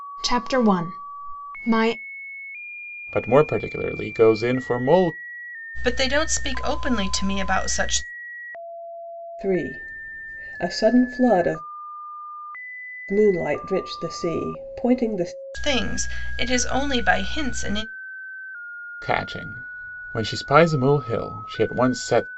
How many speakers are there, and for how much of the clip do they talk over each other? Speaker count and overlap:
4, no overlap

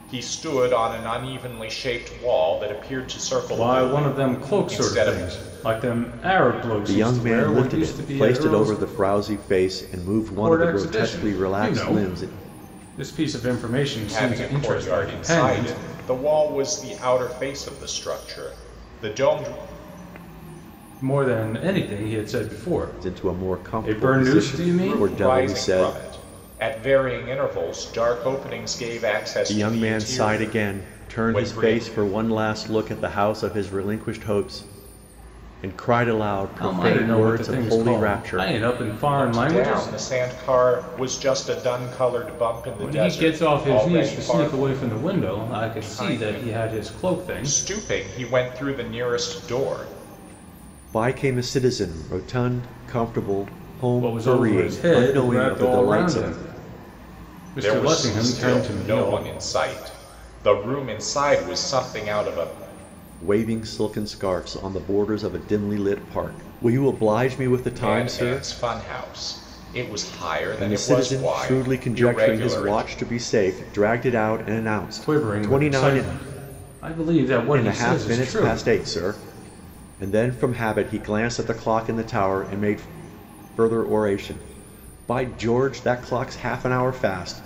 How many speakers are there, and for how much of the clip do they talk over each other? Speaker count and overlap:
3, about 33%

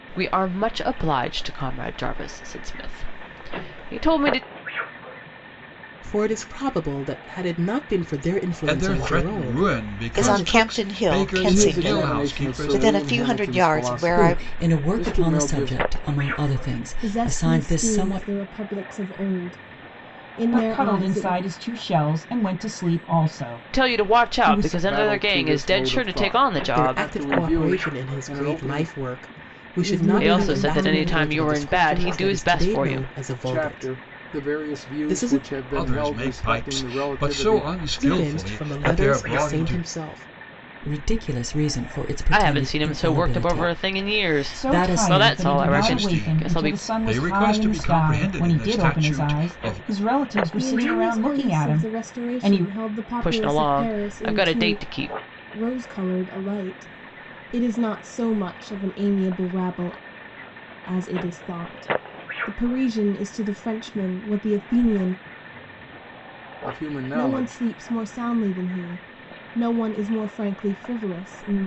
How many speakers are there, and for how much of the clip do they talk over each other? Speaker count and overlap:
8, about 50%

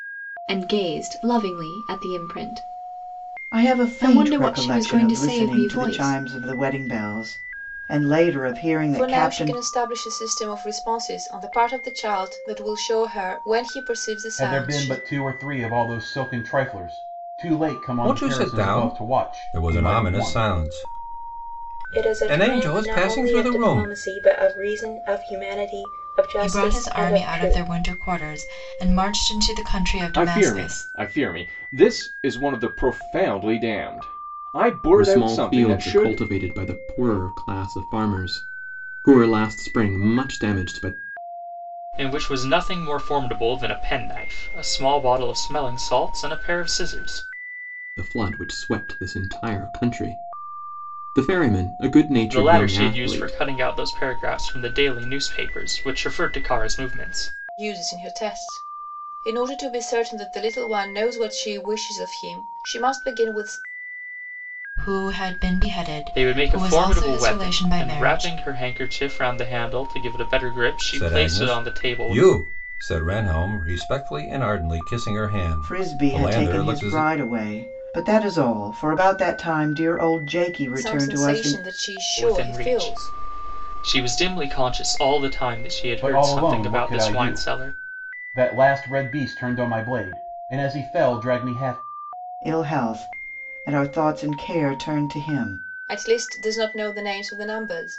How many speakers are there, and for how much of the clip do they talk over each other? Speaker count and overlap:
10, about 22%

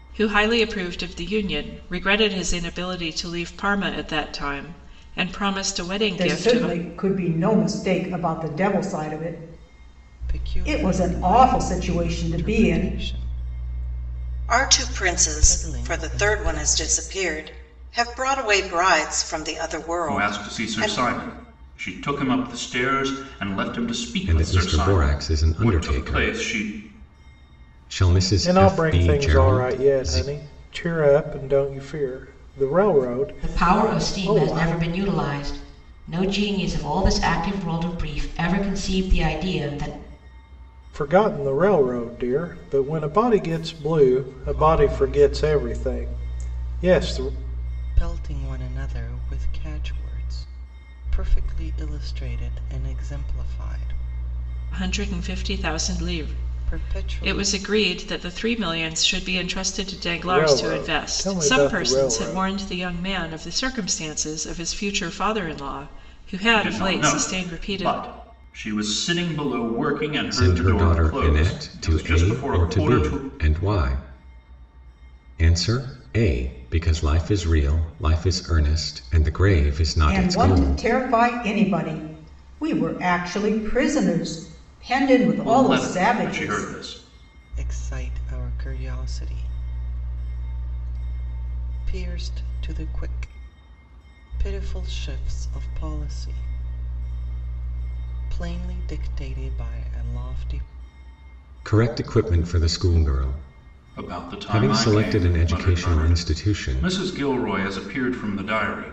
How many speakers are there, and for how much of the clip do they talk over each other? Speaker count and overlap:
8, about 28%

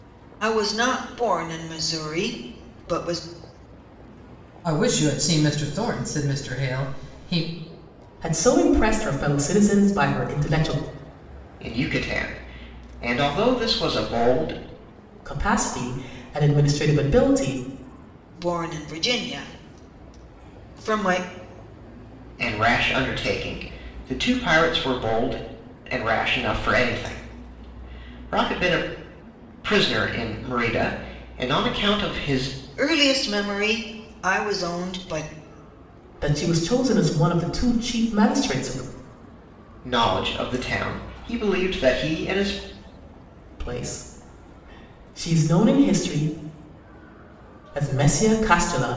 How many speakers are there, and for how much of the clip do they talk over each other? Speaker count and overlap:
4, no overlap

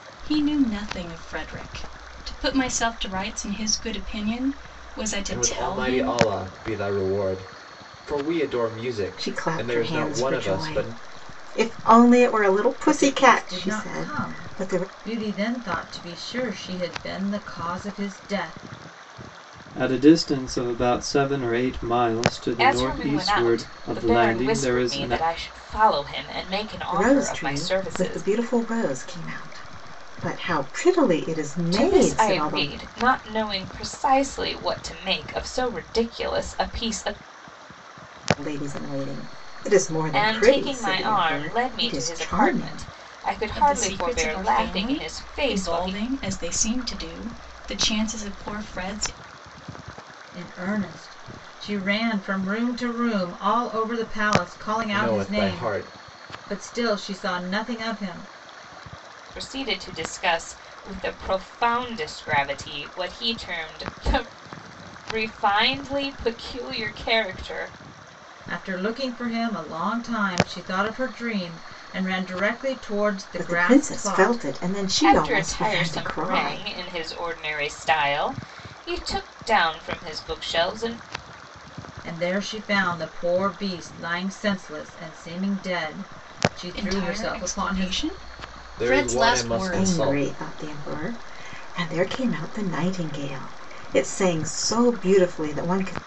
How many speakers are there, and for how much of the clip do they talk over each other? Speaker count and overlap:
6, about 23%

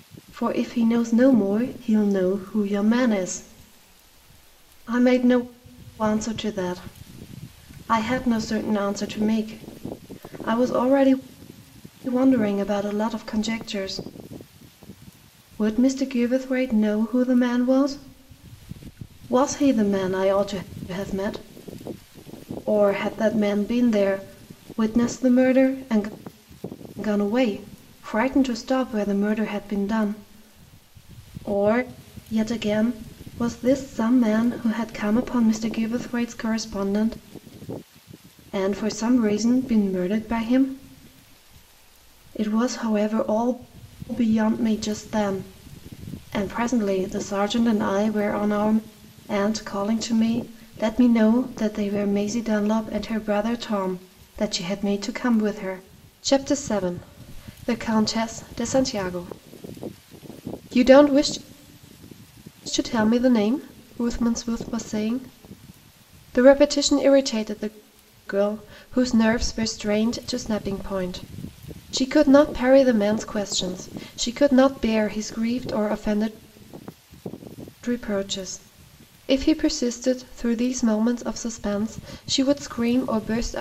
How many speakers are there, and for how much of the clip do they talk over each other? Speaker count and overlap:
1, no overlap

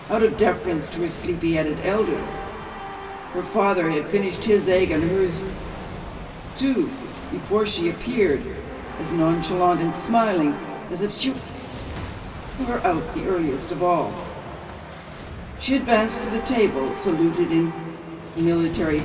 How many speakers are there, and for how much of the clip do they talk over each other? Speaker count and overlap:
1, no overlap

